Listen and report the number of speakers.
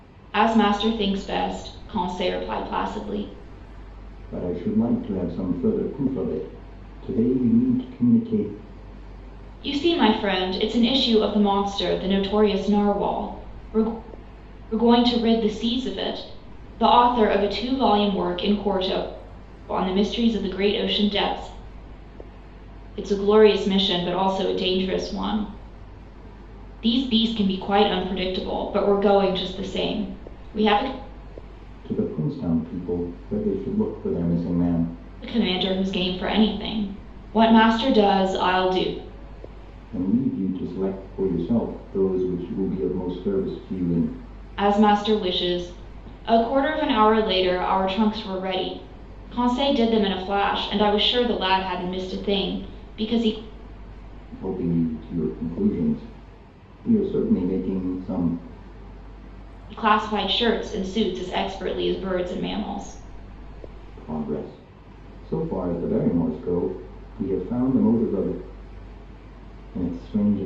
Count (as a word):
two